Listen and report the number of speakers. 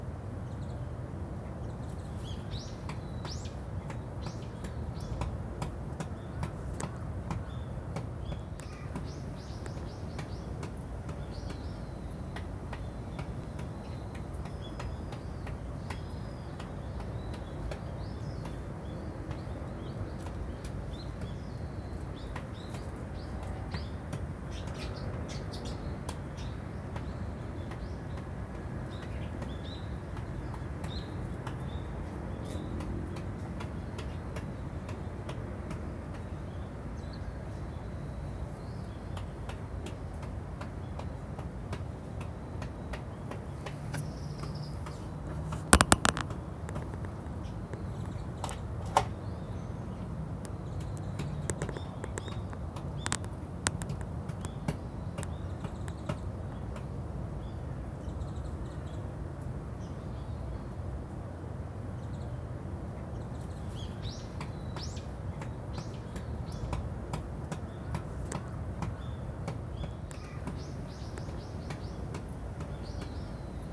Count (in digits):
0